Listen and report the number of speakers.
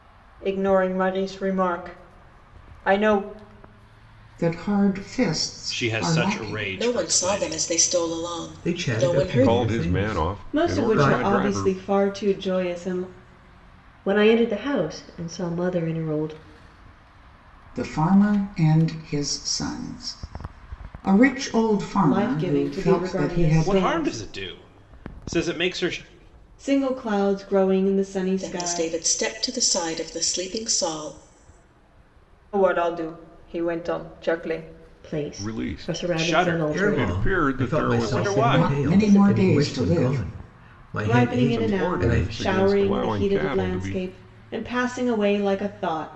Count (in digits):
8